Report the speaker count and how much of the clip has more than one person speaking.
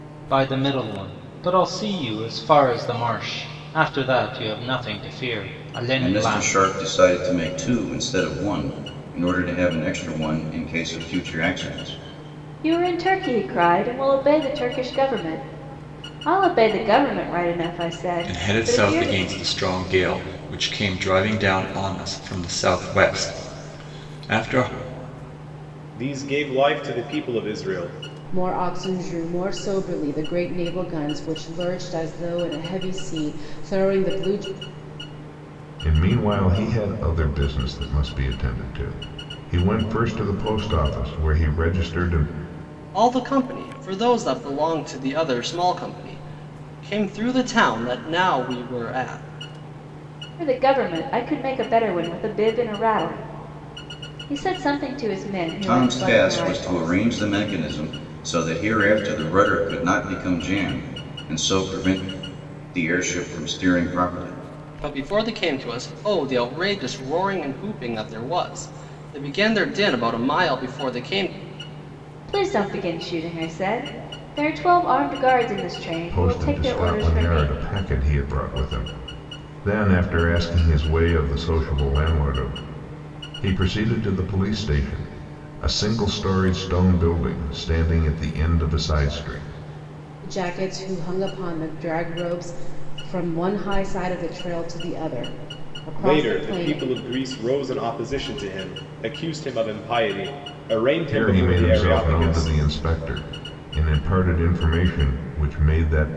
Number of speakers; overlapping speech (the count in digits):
8, about 7%